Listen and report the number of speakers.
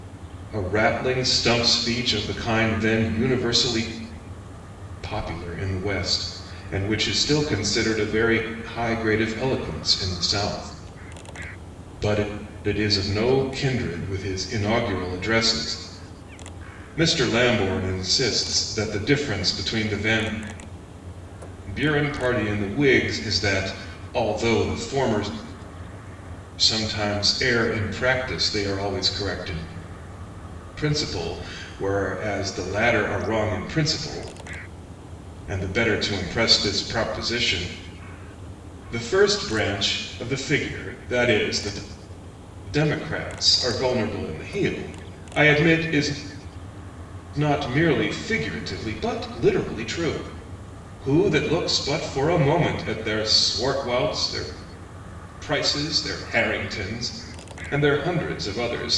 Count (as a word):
one